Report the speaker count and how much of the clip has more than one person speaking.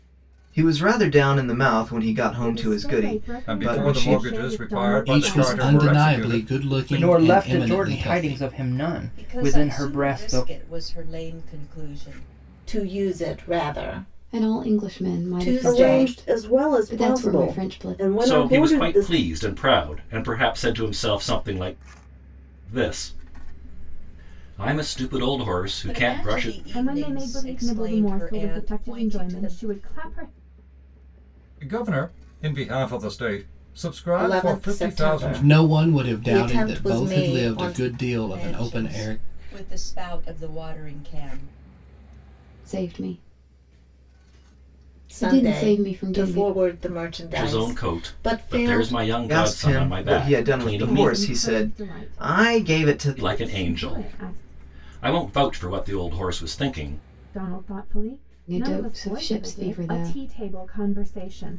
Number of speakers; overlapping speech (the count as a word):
ten, about 49%